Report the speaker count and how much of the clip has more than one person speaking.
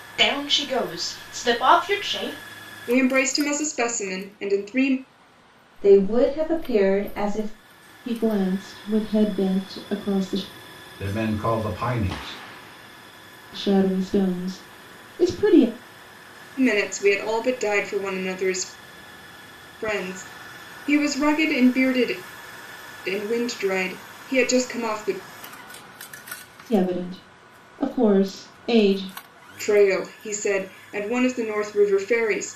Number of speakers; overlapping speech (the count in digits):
5, no overlap